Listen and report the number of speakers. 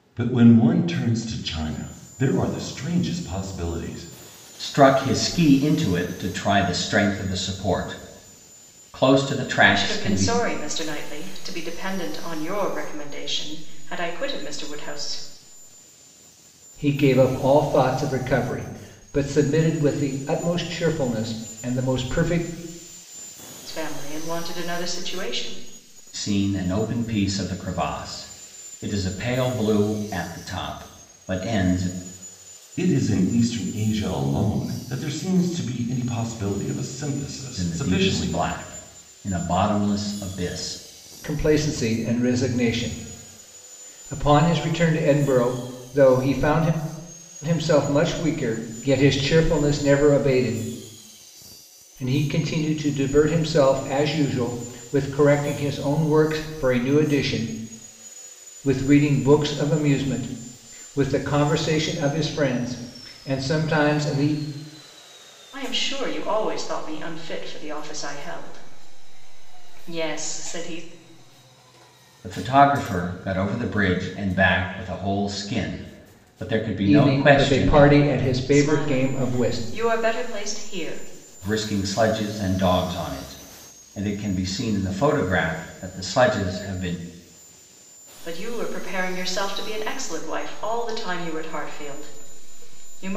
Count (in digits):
4